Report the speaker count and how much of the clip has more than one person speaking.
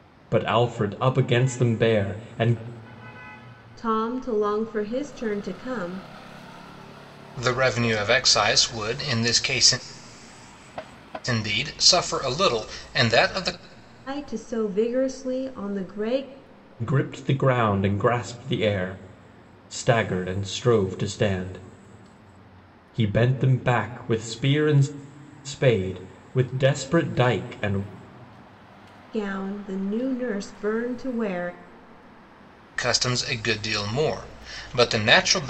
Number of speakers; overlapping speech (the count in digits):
3, no overlap